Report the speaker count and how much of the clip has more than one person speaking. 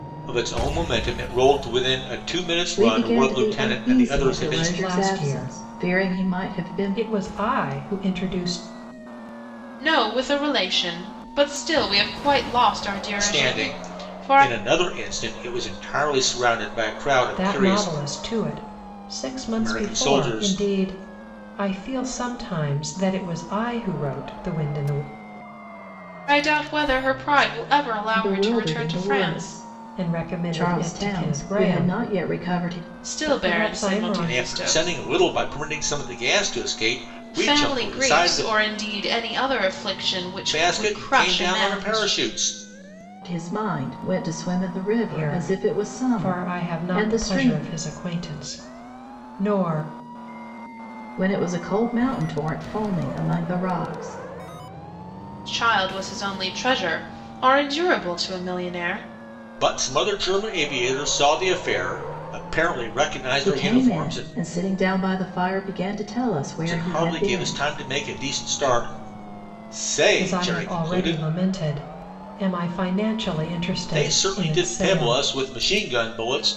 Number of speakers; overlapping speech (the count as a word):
four, about 30%